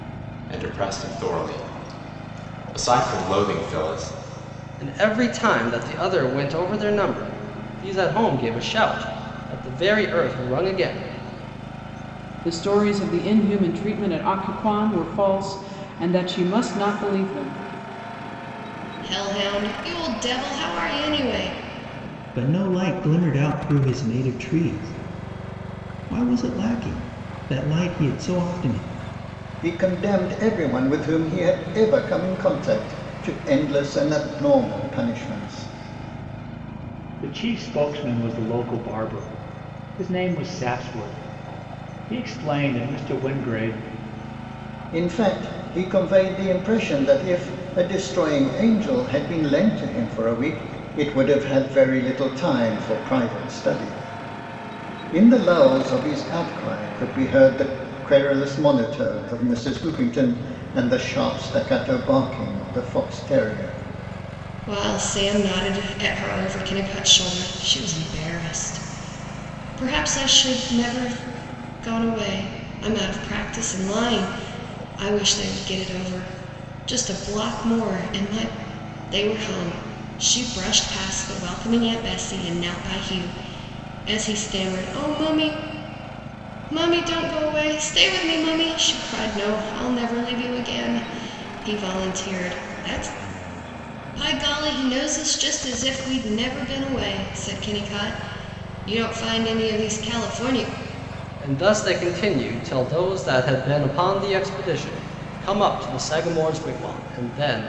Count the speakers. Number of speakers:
7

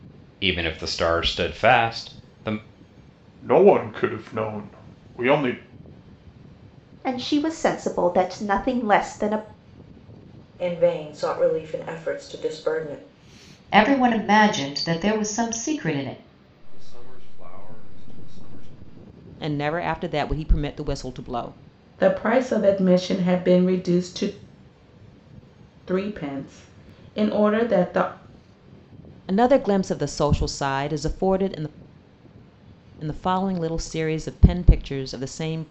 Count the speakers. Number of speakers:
8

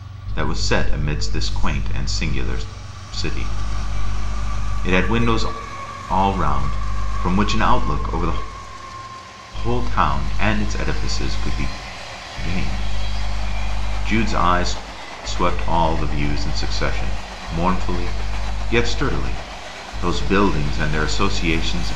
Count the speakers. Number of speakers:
1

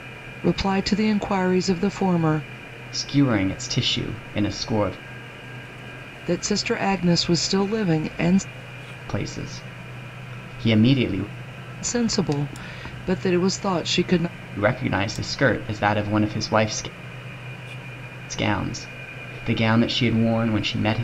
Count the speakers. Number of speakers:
2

